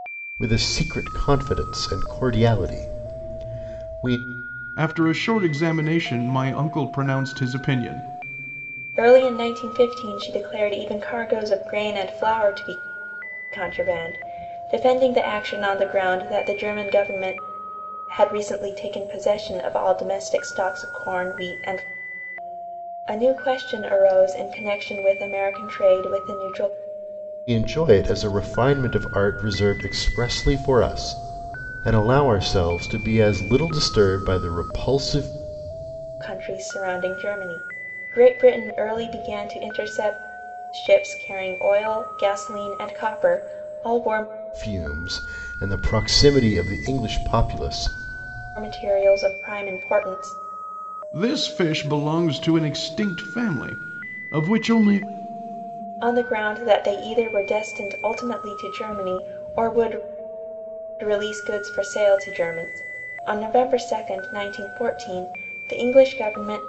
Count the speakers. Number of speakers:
3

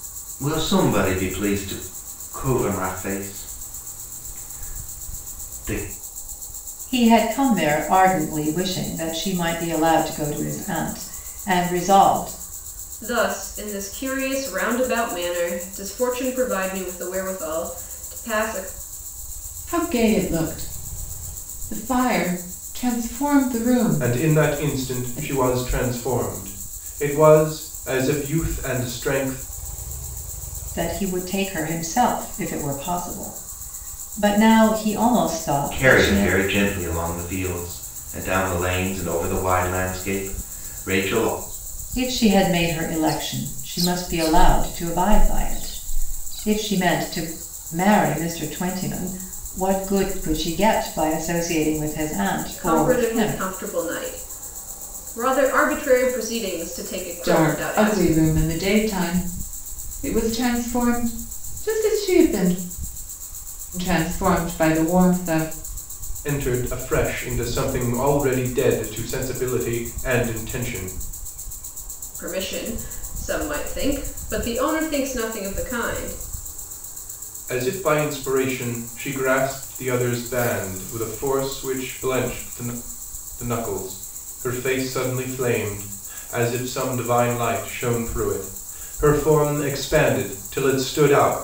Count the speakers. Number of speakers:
5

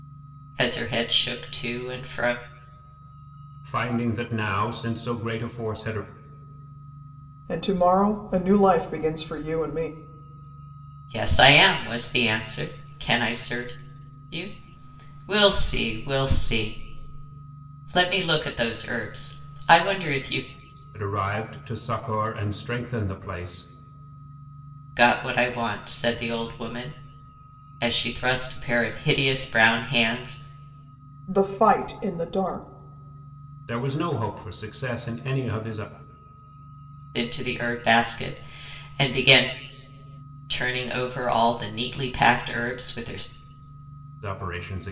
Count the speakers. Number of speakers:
3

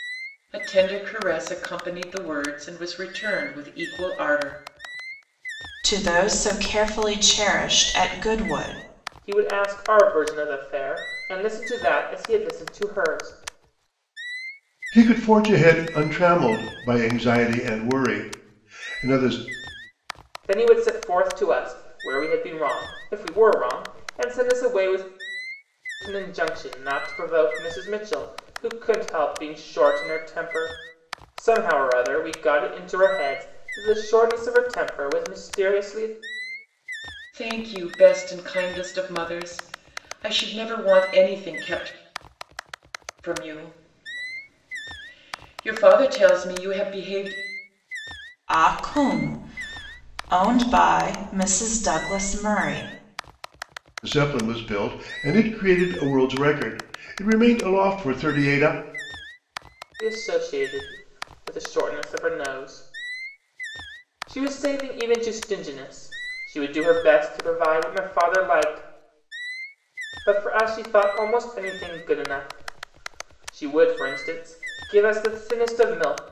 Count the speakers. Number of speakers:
4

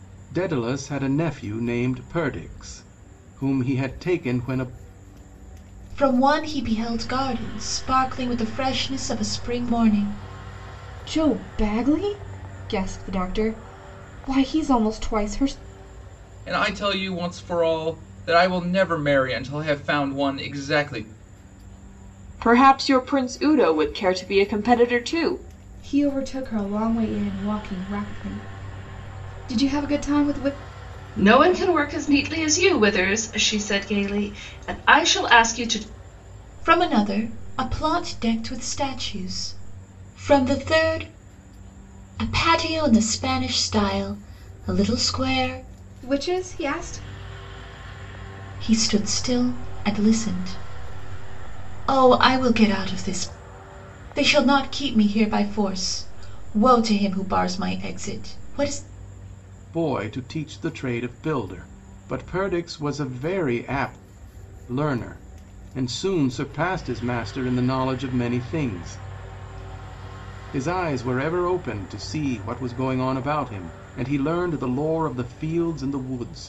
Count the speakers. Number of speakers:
7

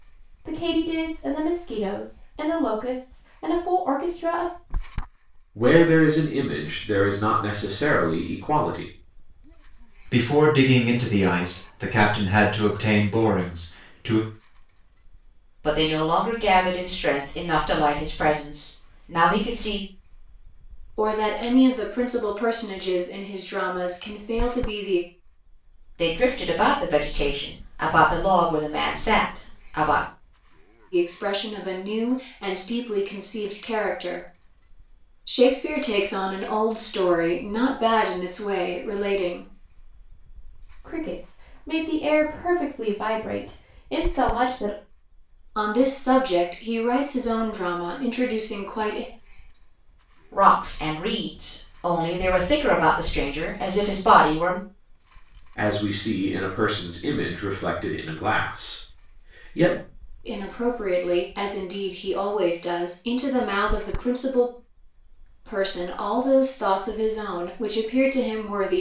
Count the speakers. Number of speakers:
5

